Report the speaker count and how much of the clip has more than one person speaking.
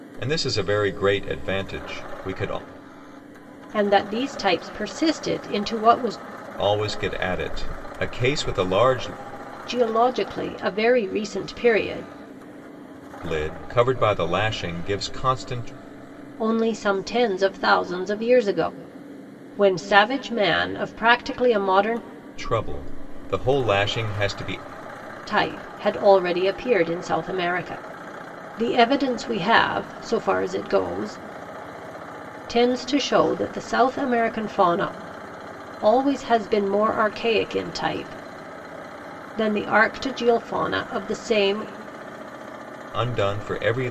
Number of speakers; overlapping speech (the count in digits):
2, no overlap